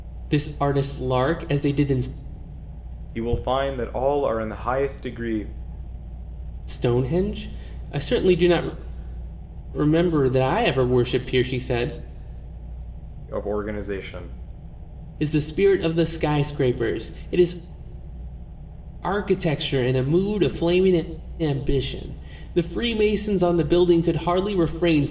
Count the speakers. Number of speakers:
two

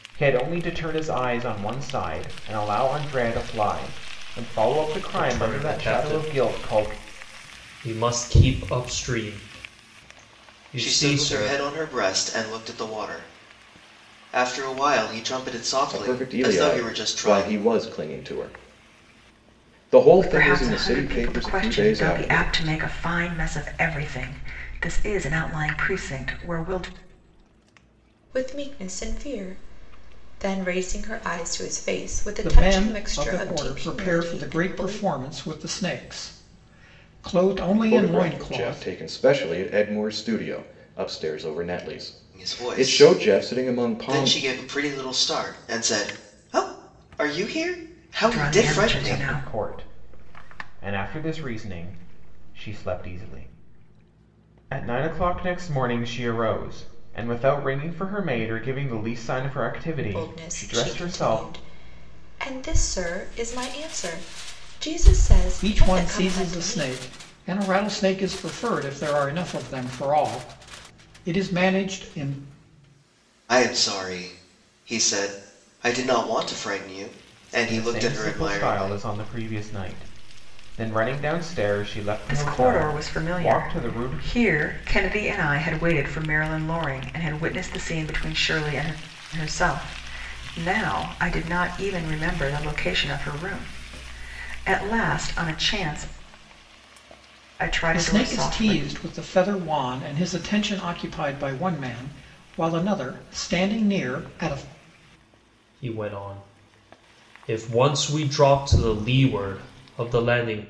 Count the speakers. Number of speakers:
seven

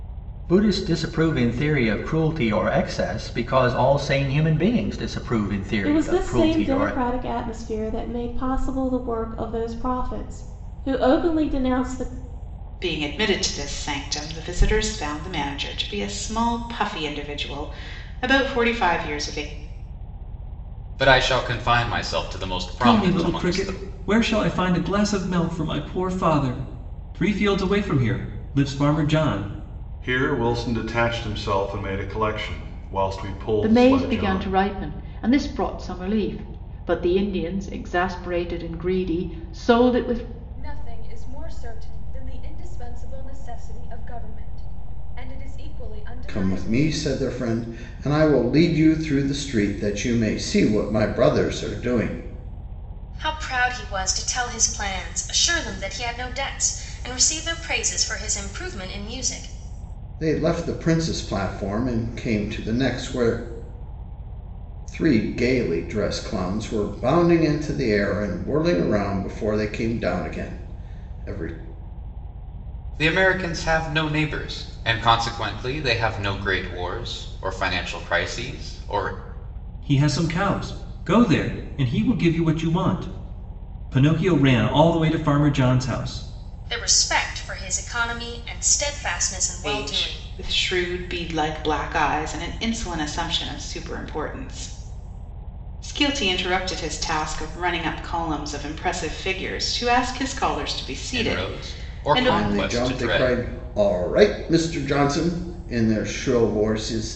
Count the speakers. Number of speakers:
ten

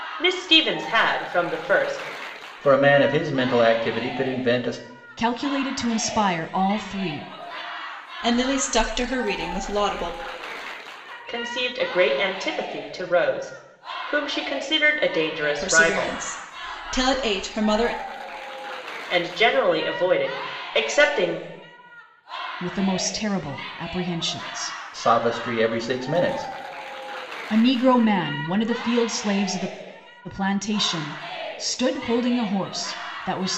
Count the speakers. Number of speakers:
four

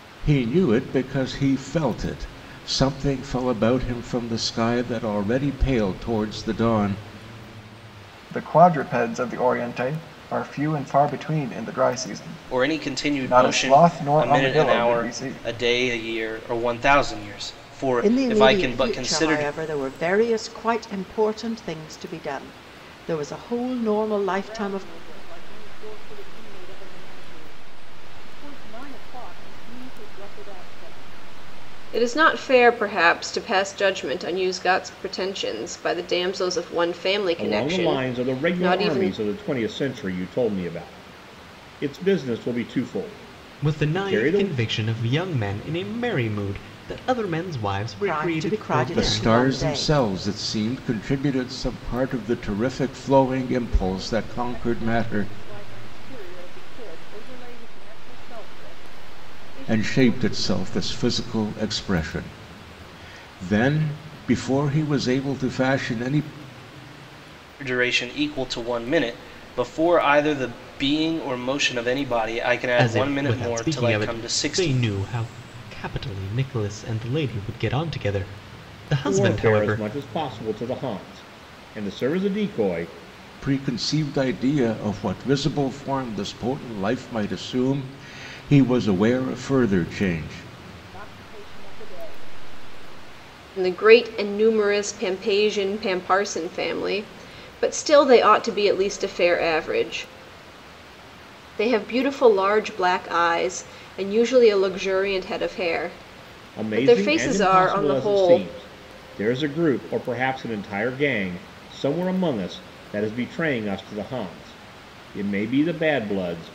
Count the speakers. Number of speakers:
eight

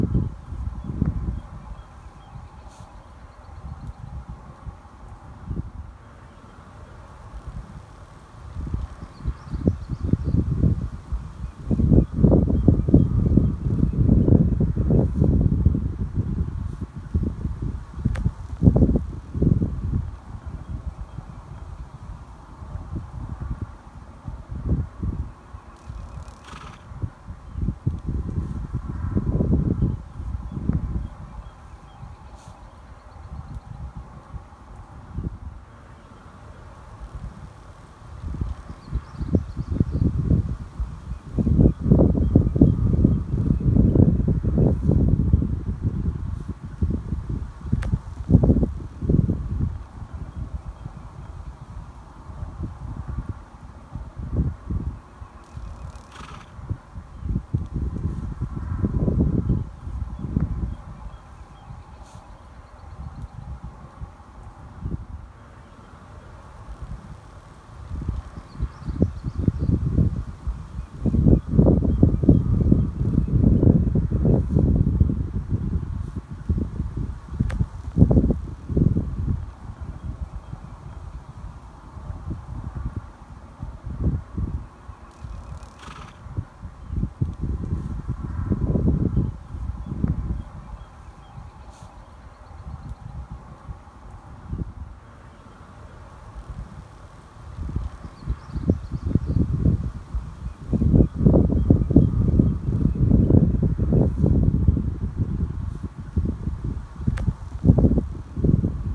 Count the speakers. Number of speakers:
zero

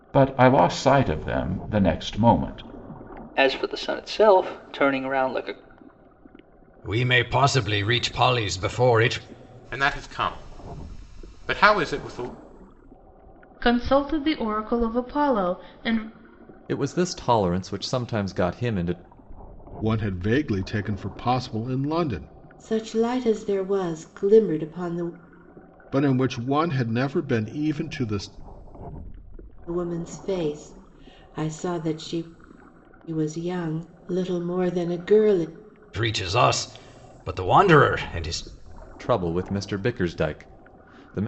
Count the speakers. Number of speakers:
eight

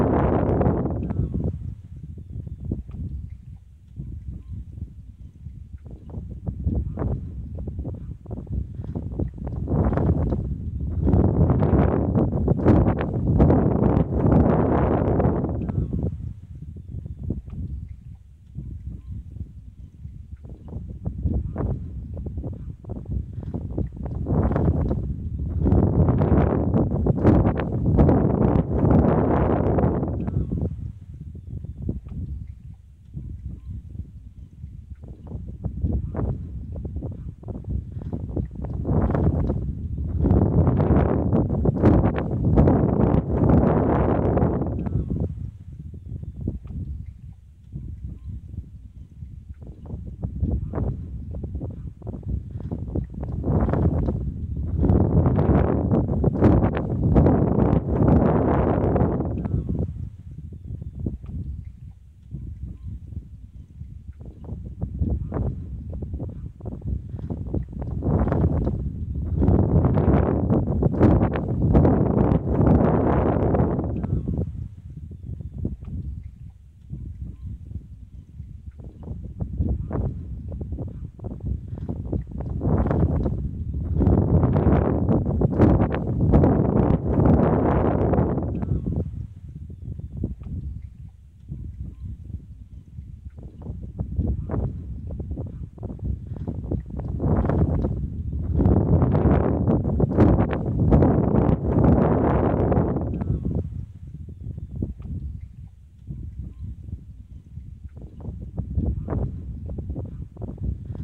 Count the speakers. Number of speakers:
zero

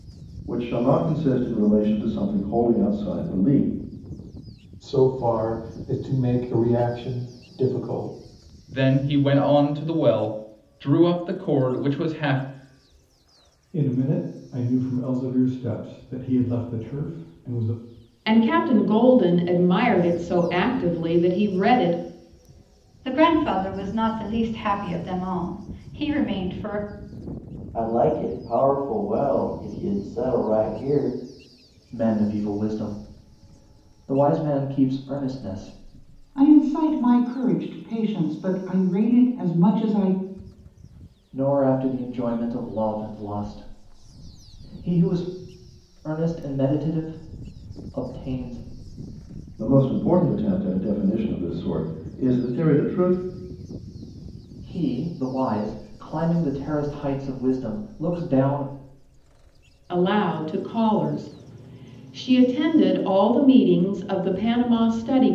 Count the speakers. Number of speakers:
nine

